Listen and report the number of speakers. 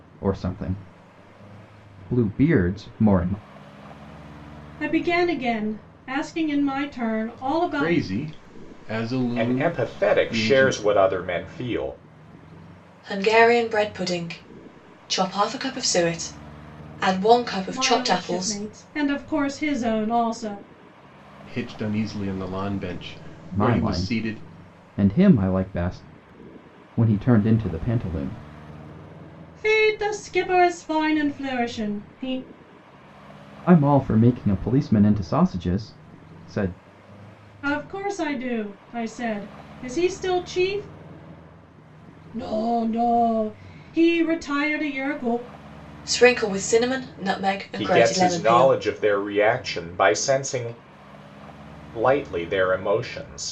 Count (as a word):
five